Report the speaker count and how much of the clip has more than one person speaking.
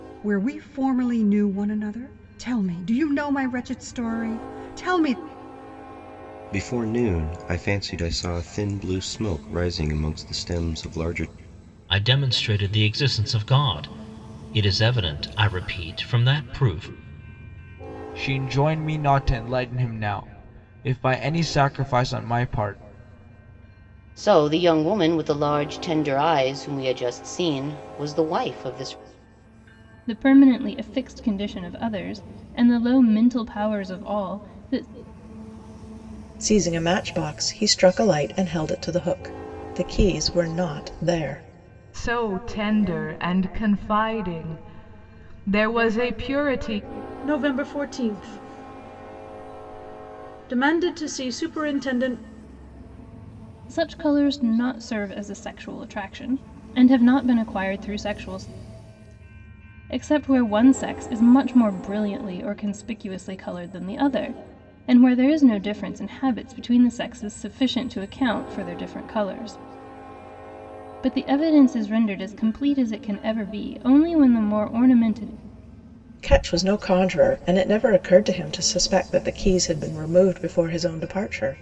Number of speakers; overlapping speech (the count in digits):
9, no overlap